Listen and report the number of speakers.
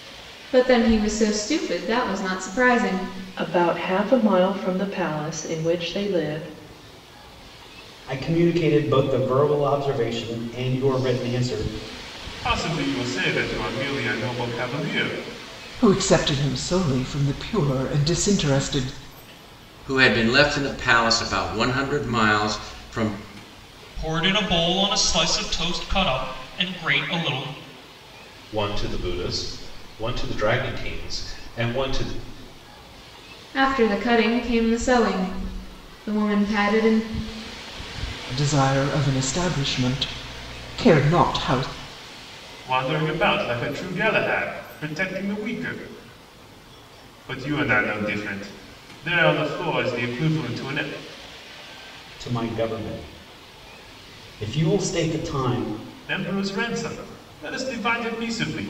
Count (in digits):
8